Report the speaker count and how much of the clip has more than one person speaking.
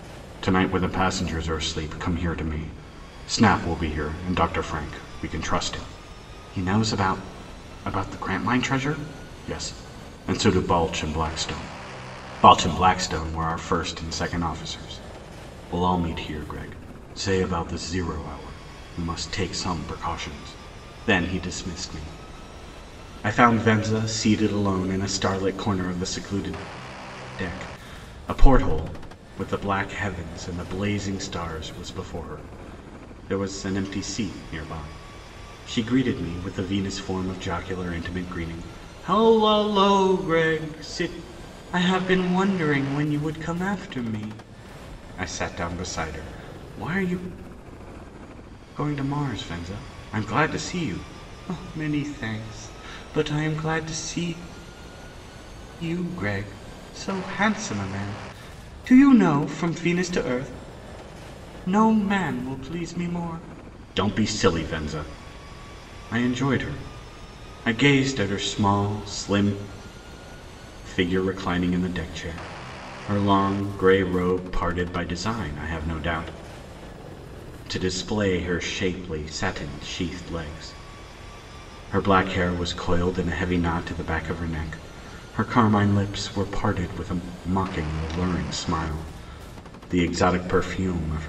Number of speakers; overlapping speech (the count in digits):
1, no overlap